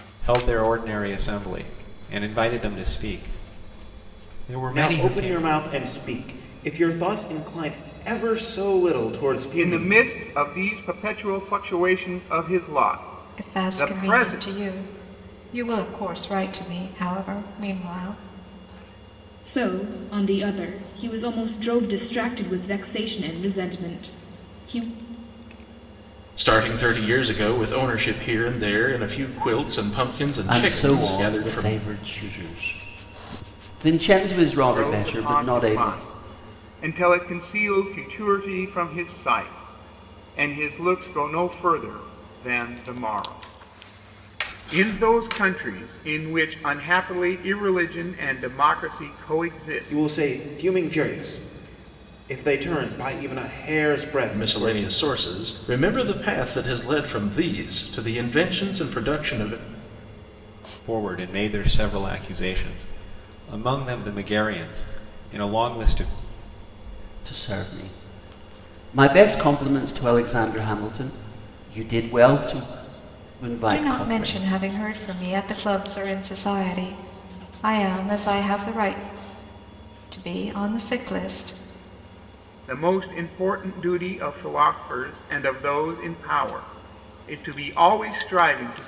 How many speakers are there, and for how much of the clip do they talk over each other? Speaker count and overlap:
7, about 8%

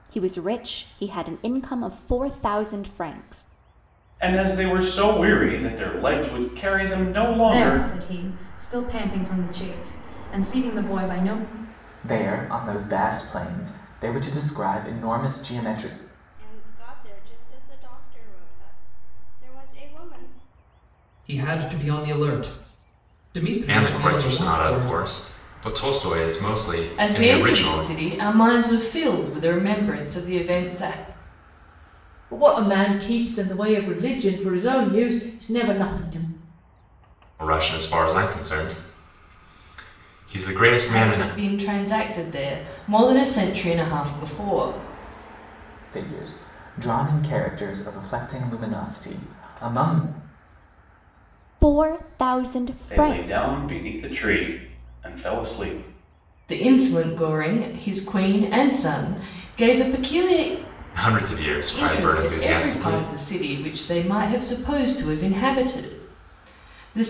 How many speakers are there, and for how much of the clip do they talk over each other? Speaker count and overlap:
9, about 8%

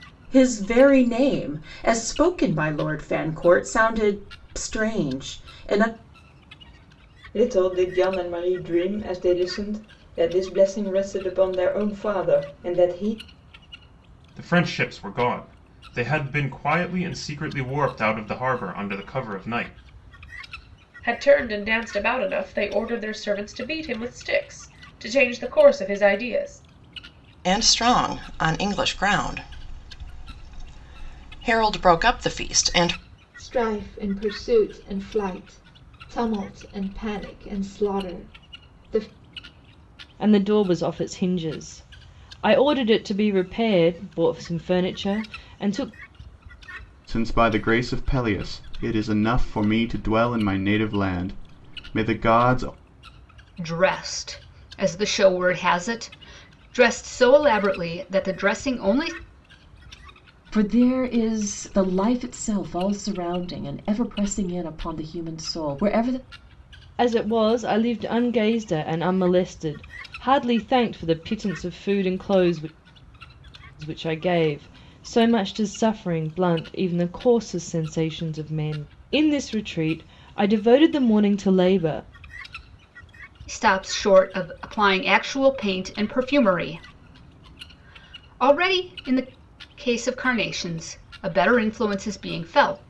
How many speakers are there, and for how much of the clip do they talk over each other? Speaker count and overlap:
10, no overlap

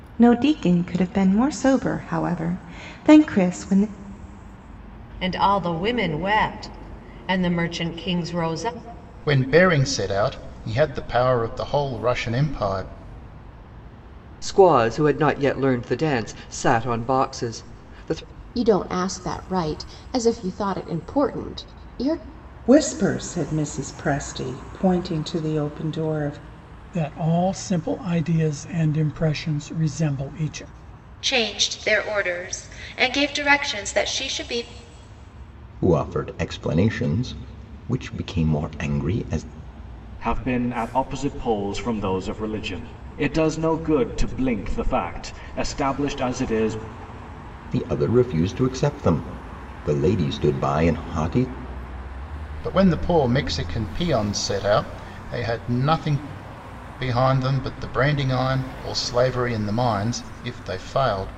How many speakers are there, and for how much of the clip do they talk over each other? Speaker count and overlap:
10, no overlap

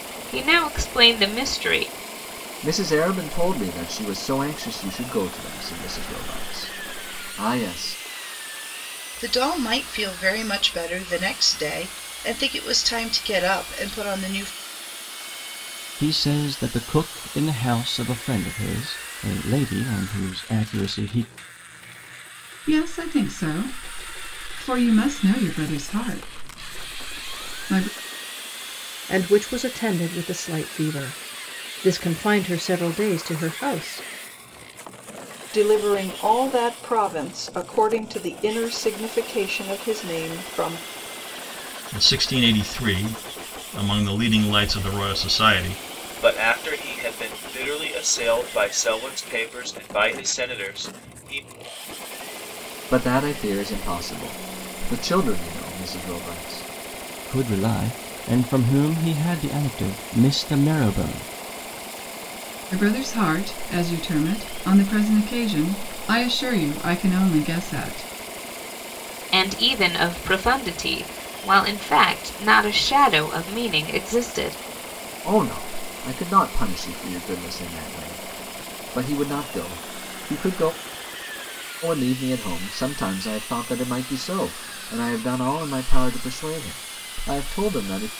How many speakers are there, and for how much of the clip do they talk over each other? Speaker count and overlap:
9, no overlap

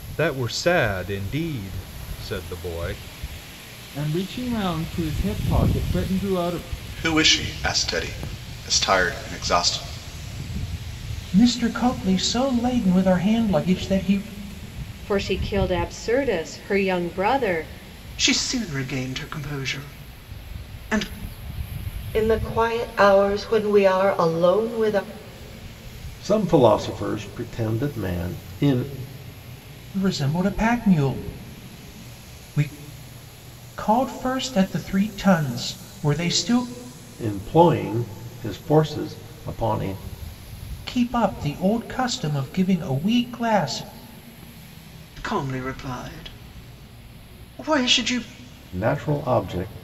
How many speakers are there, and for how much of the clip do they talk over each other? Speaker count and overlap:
8, no overlap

